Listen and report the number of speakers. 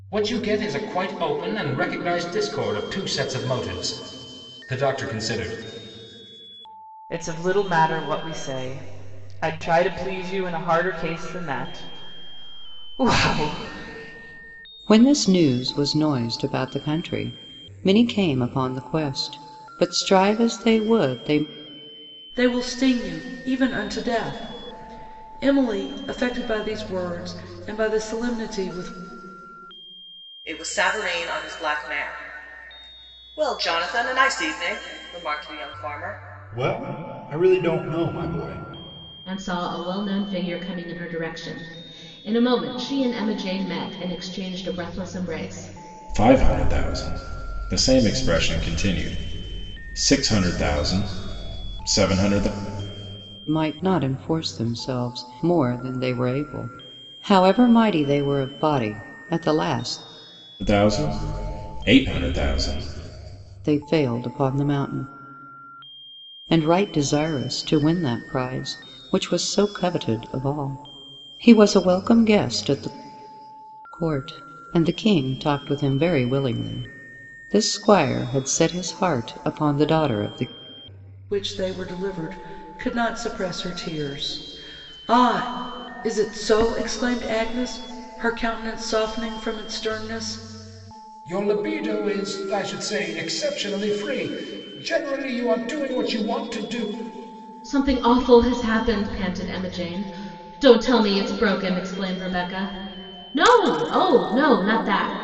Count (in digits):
8